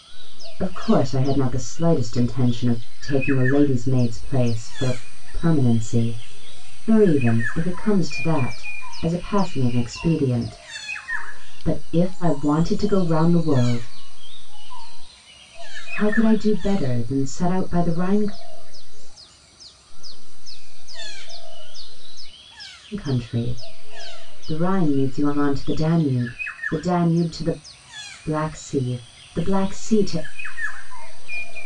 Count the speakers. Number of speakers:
two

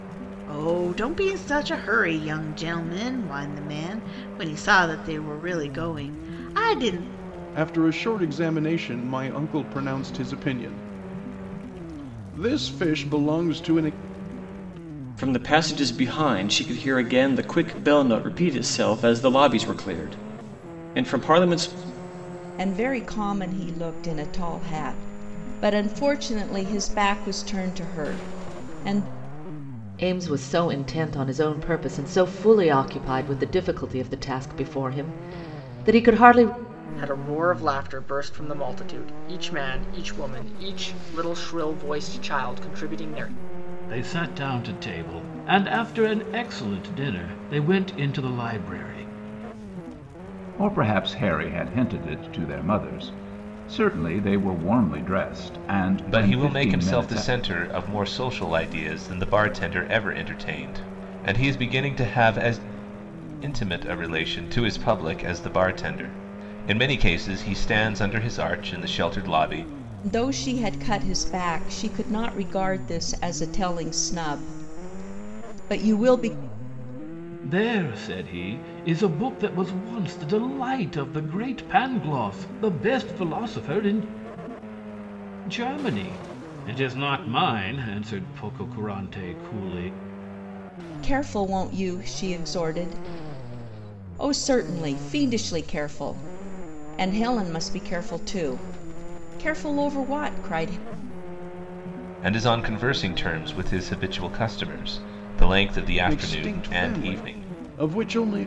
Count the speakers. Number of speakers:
nine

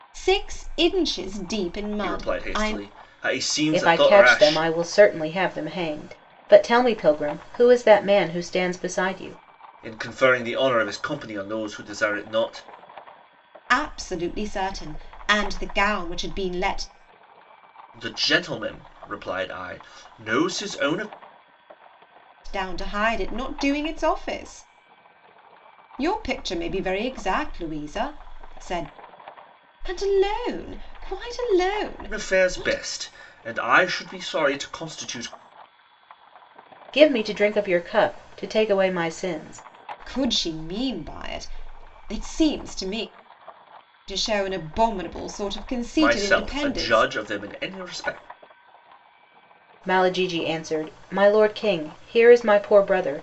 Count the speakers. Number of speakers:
three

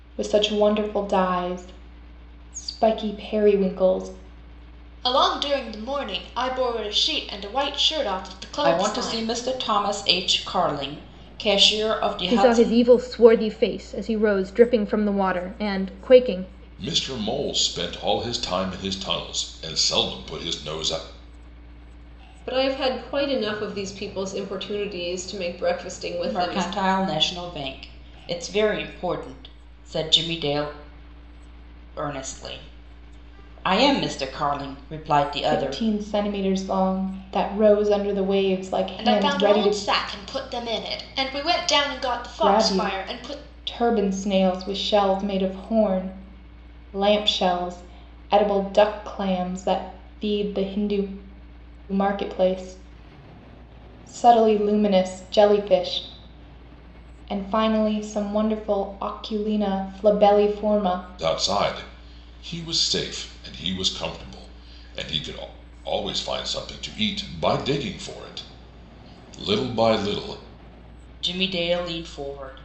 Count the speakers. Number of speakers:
six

